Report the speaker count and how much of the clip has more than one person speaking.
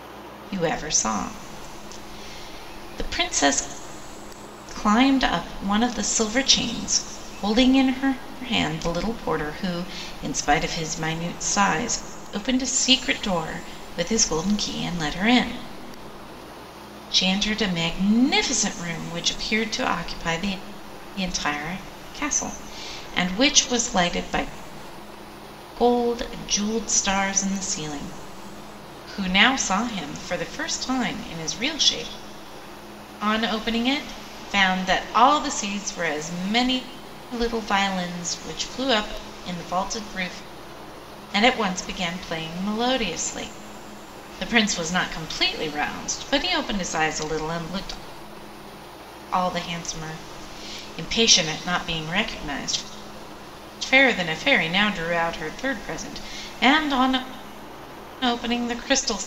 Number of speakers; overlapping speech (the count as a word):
one, no overlap